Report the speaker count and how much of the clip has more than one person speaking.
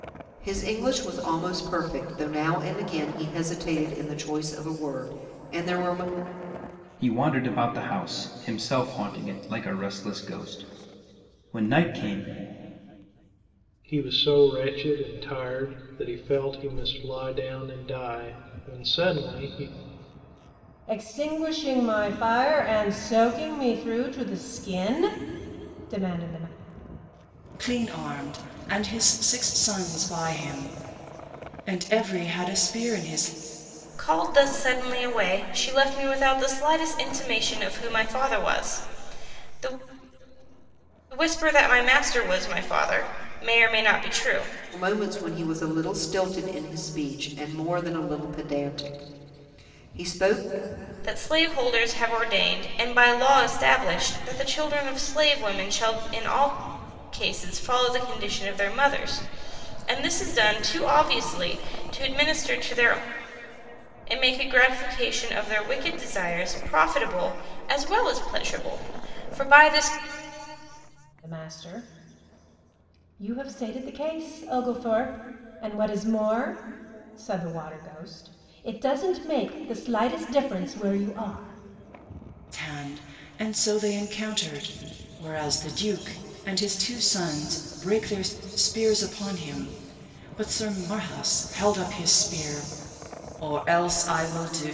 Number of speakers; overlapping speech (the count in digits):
6, no overlap